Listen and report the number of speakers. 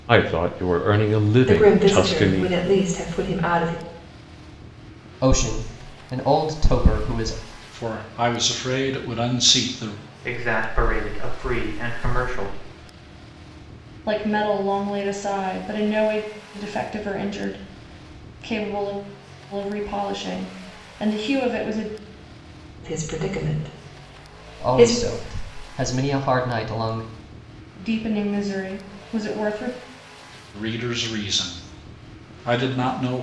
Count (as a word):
six